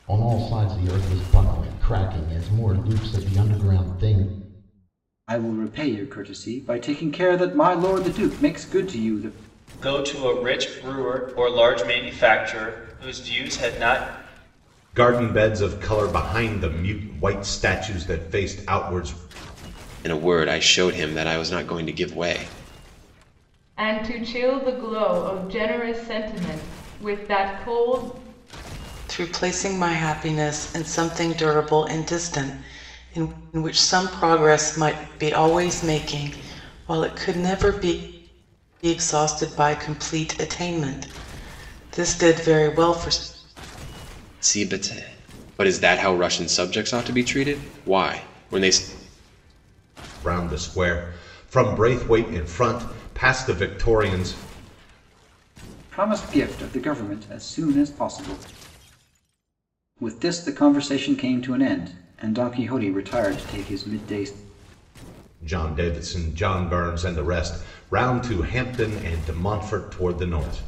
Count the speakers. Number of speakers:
7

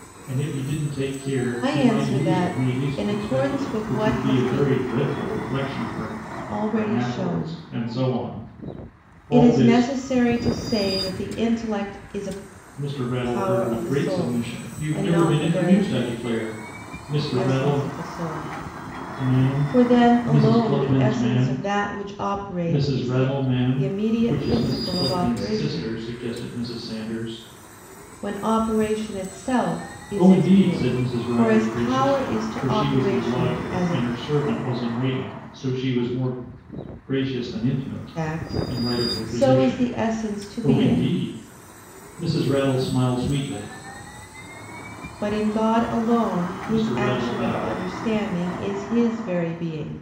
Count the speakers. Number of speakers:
2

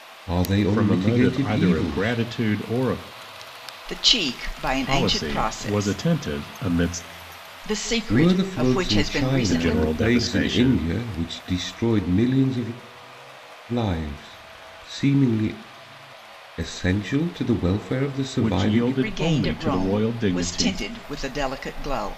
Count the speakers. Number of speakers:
3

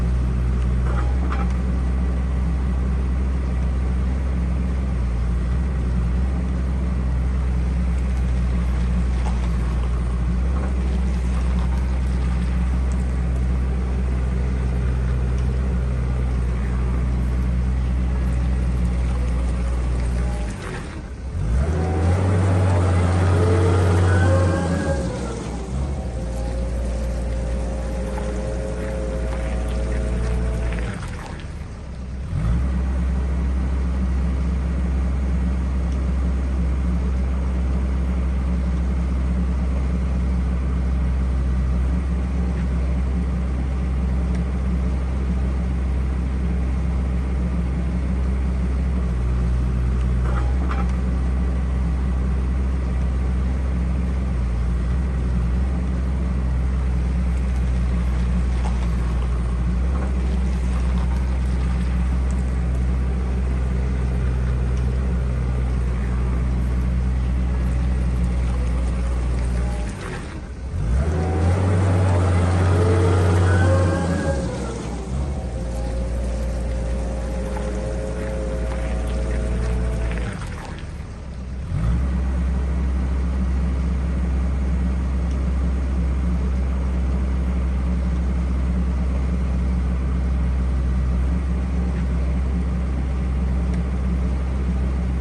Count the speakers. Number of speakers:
0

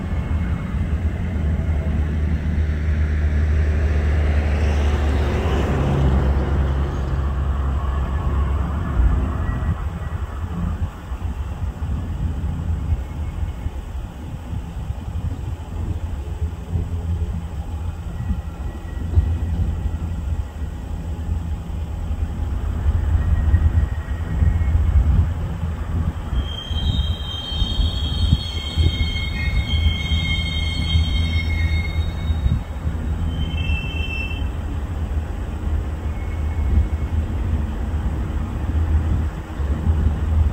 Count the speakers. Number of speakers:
0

